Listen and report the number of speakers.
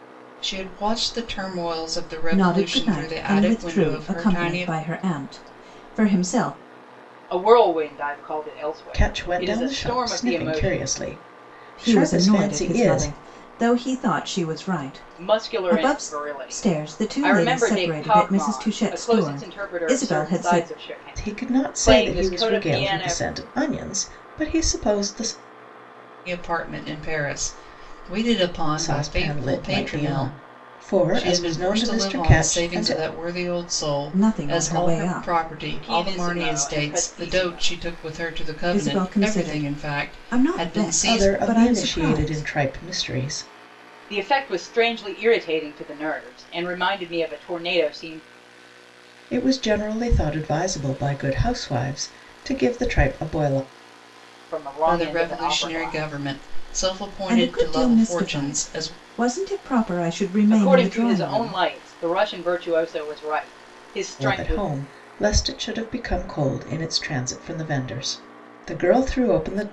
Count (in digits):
4